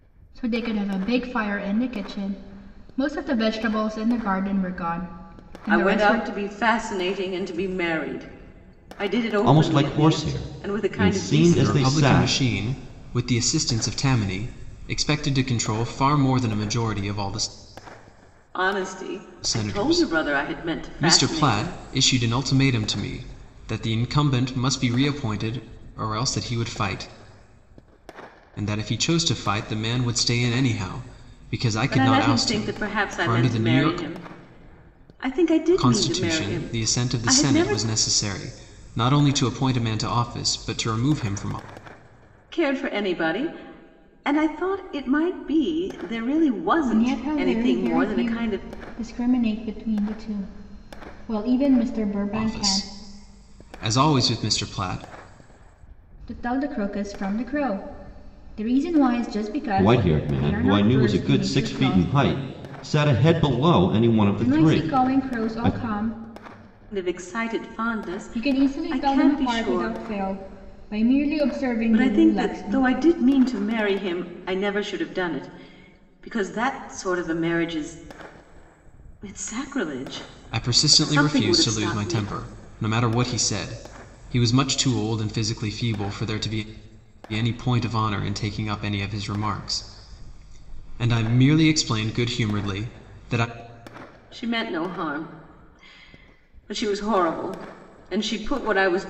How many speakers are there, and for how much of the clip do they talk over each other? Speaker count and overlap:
4, about 22%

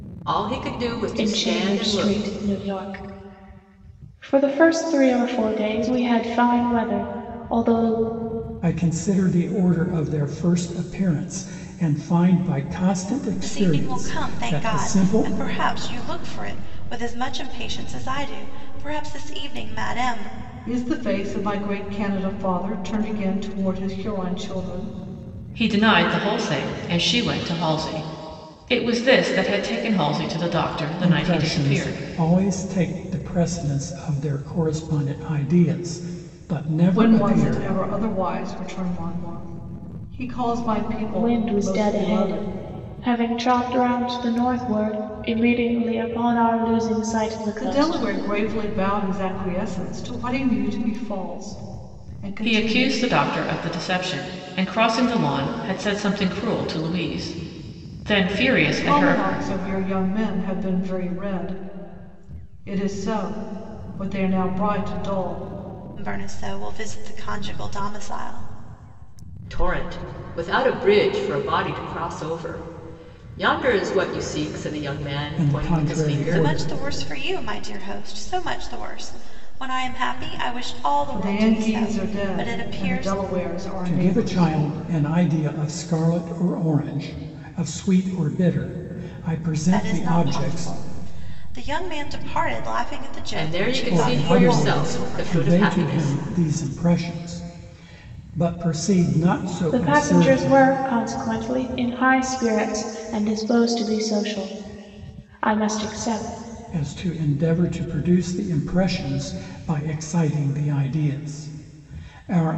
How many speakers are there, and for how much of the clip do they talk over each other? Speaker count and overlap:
6, about 16%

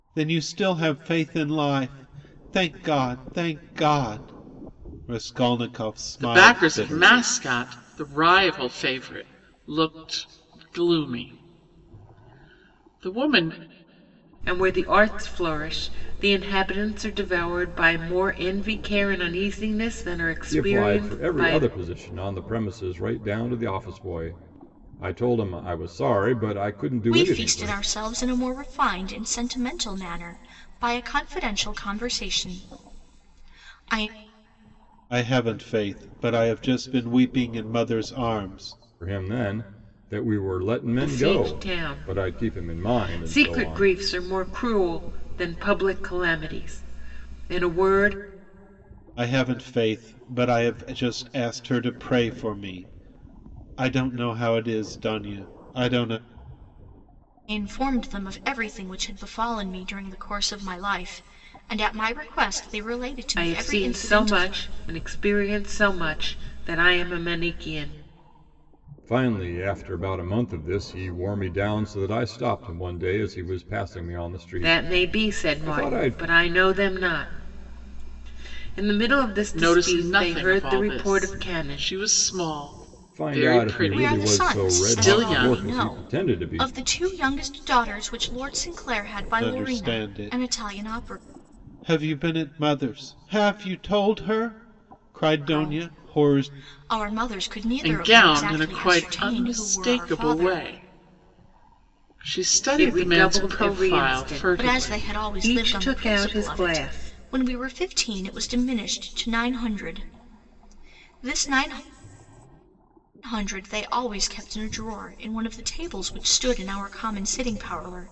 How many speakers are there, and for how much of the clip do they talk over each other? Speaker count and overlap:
5, about 21%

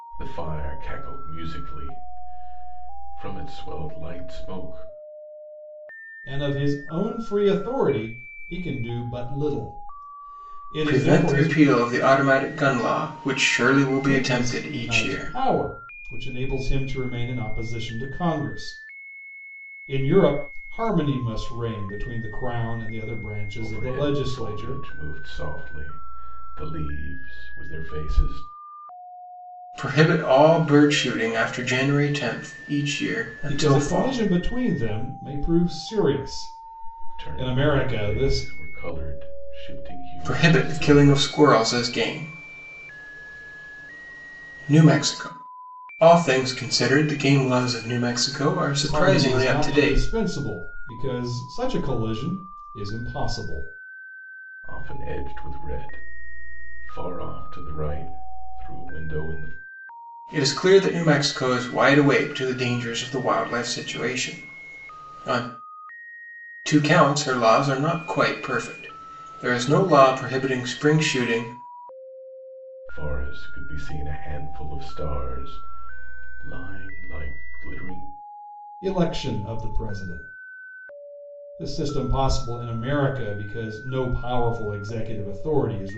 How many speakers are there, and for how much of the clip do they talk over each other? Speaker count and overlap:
3, about 9%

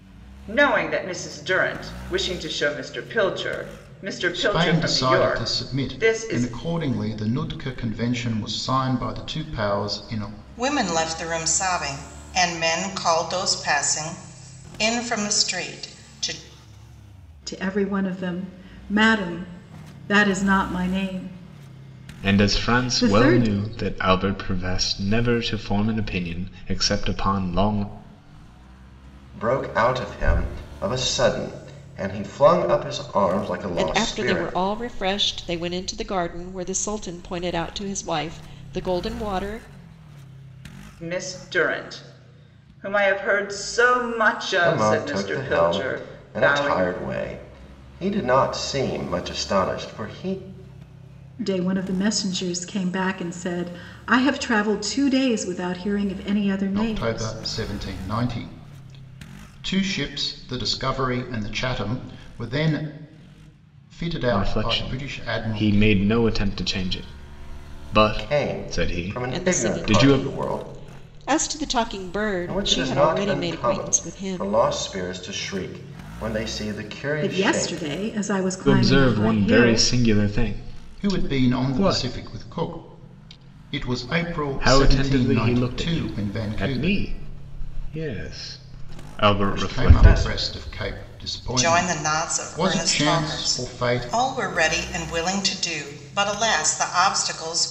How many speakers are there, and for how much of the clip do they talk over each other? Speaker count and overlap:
7, about 24%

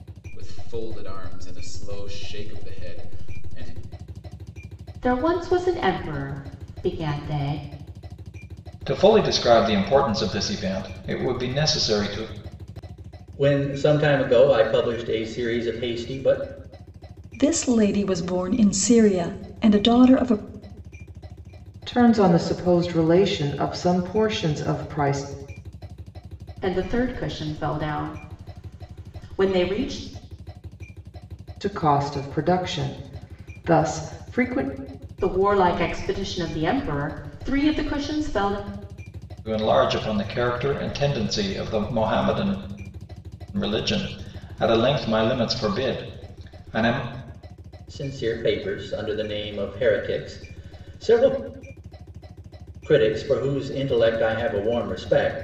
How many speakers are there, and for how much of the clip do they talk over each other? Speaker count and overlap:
6, no overlap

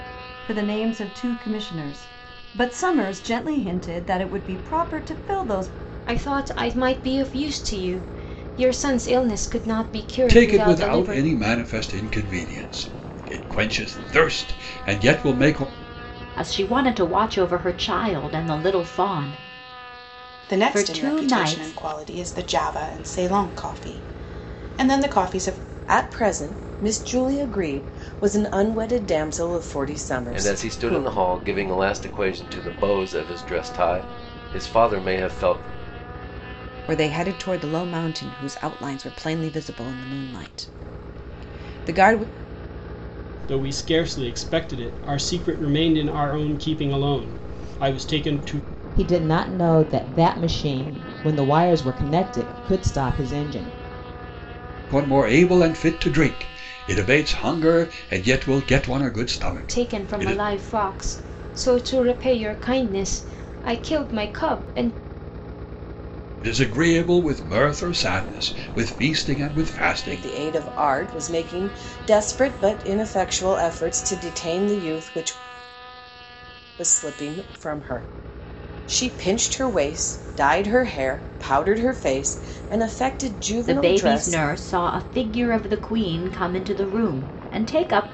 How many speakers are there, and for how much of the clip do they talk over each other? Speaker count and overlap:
10, about 6%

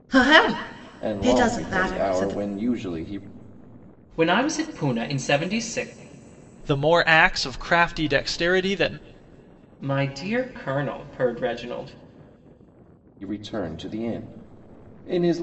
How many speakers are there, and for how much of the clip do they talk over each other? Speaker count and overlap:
4, about 10%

